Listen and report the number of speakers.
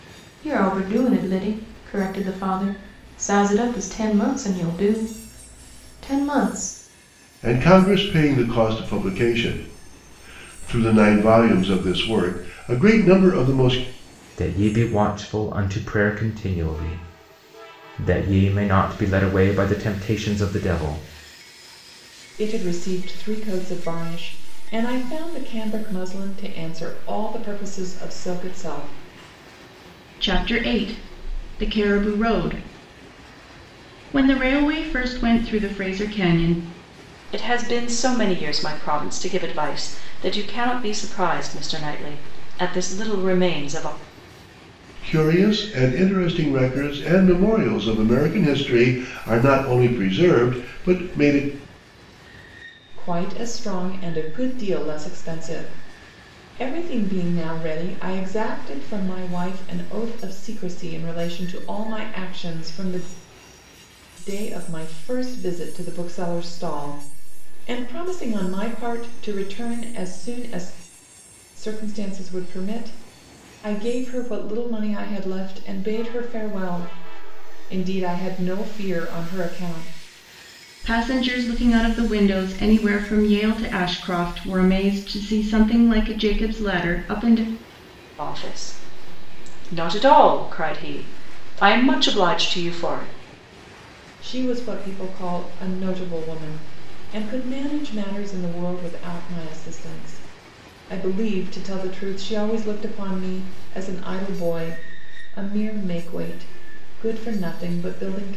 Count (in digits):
6